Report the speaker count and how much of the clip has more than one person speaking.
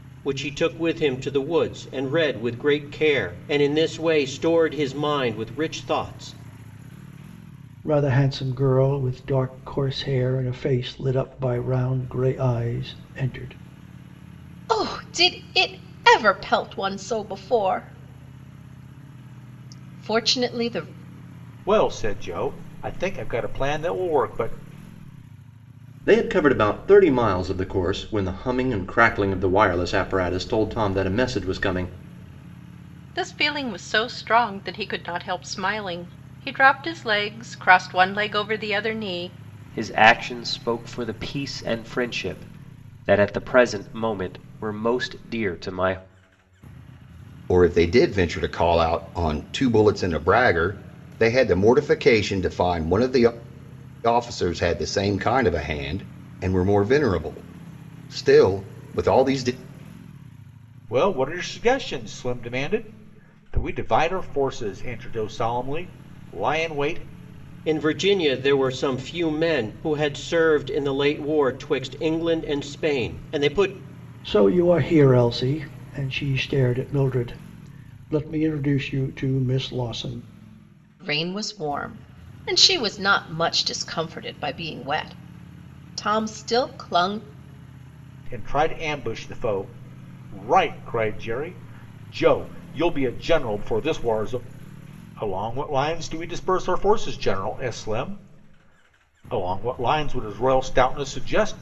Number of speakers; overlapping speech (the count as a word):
eight, no overlap